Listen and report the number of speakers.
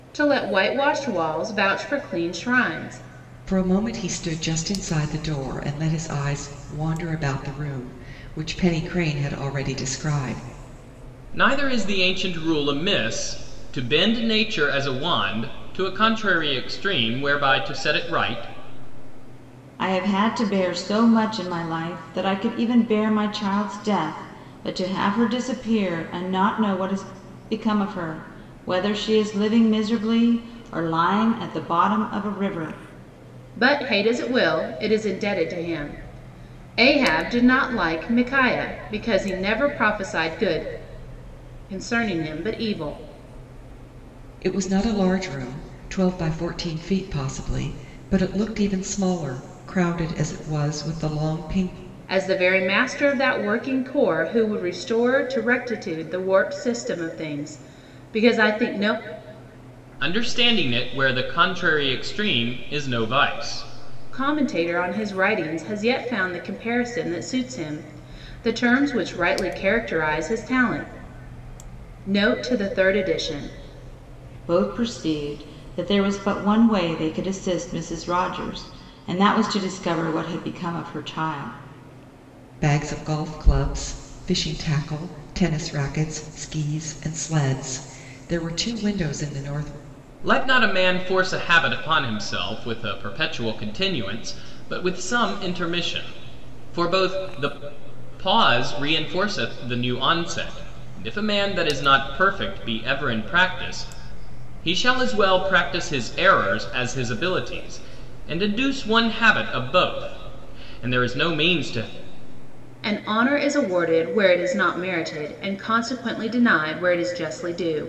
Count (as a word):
four